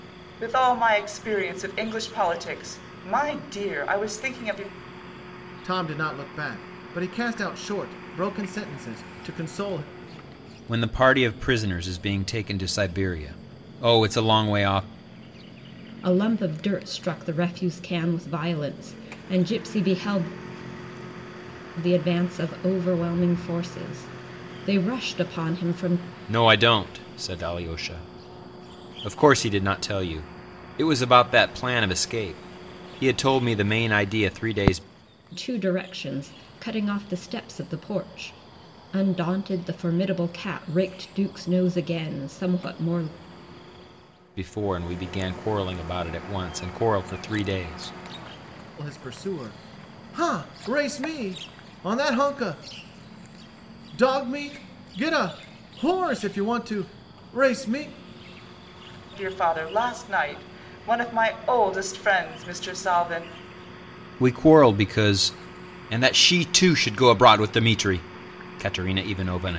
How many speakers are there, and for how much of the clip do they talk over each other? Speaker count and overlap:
four, no overlap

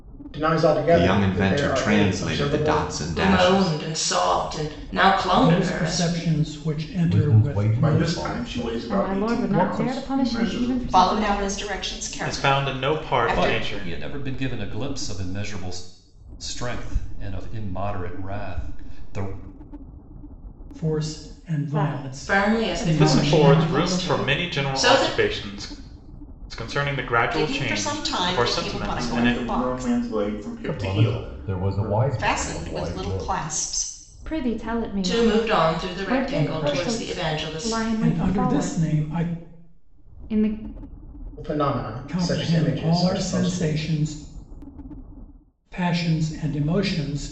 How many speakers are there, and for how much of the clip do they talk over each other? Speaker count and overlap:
ten, about 52%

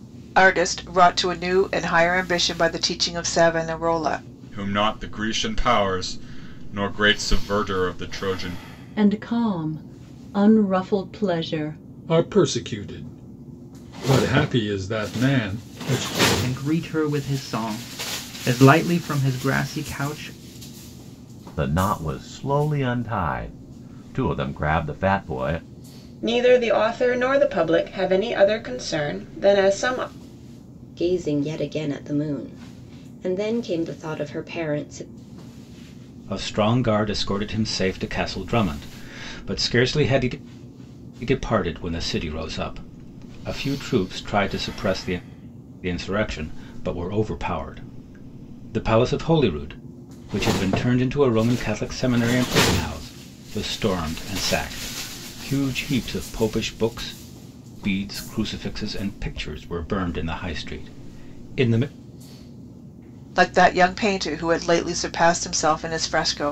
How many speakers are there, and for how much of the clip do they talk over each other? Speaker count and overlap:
nine, no overlap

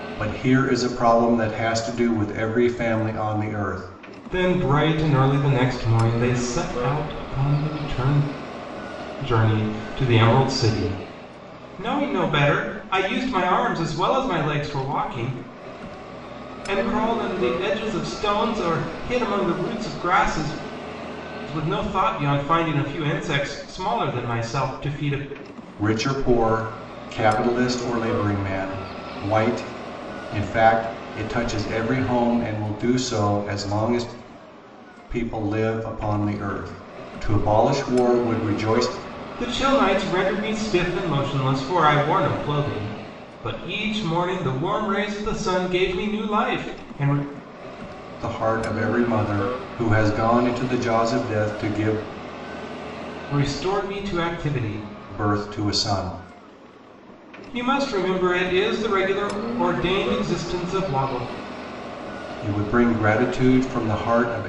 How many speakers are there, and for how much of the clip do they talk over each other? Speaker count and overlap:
two, no overlap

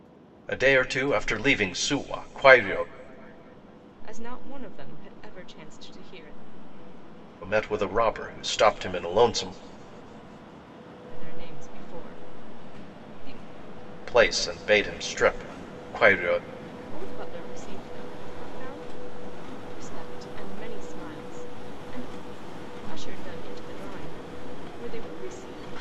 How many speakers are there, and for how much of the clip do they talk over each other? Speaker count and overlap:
two, no overlap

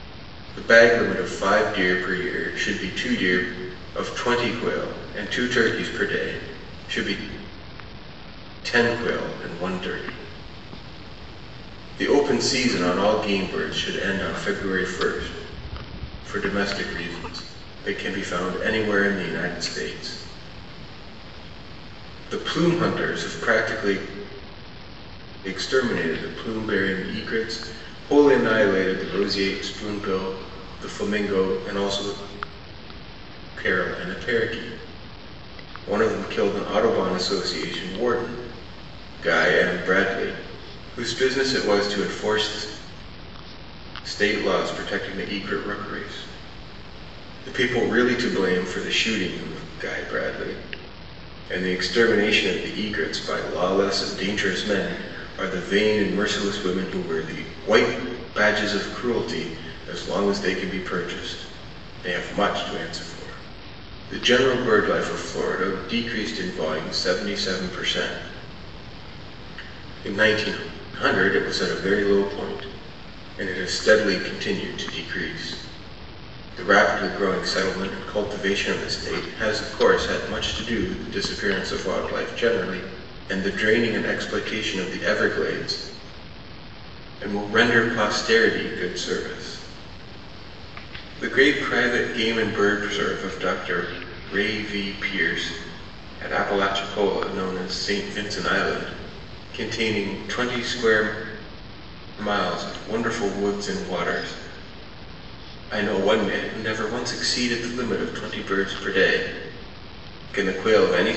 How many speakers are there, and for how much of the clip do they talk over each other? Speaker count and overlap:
one, no overlap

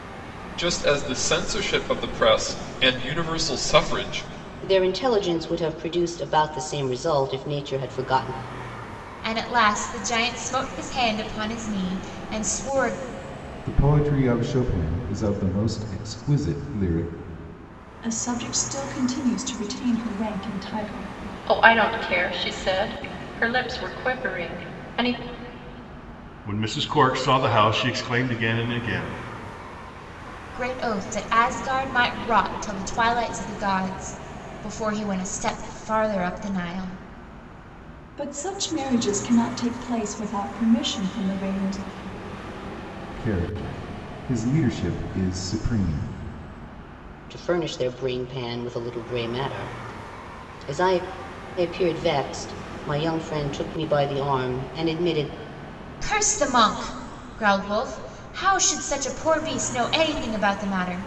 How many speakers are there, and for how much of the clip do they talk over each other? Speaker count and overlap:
seven, no overlap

